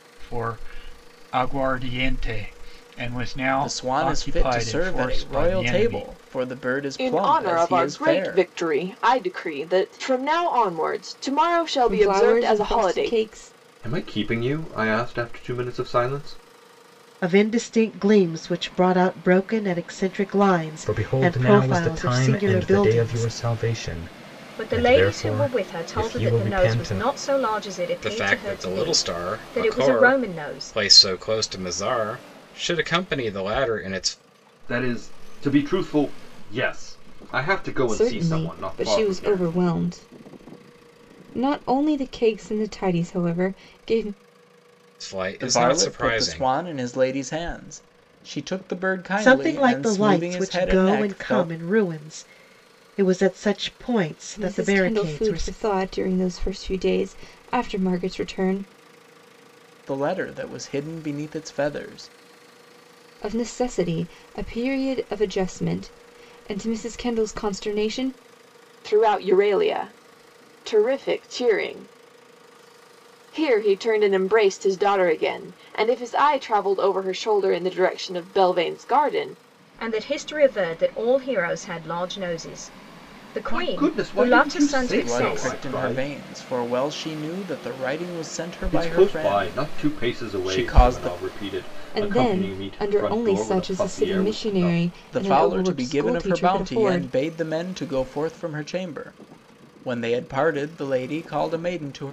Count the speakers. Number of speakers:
9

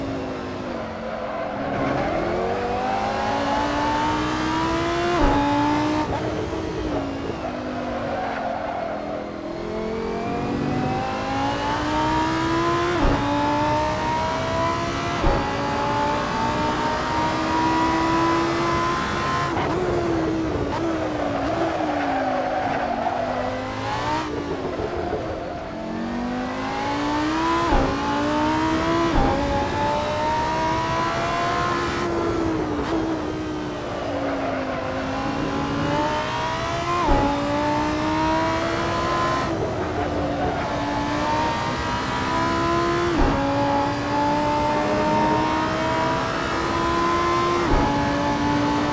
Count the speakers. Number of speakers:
0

